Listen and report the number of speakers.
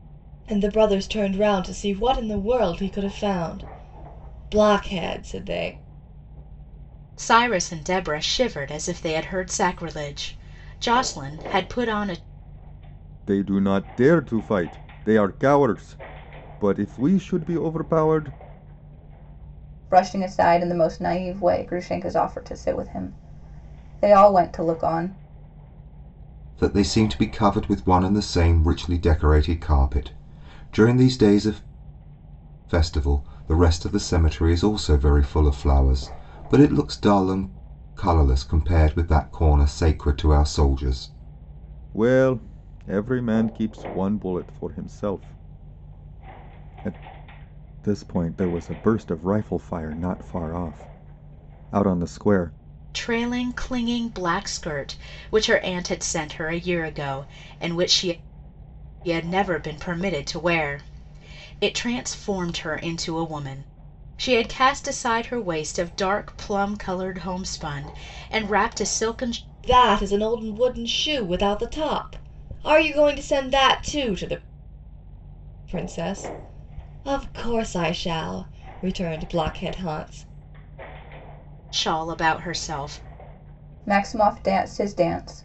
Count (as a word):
five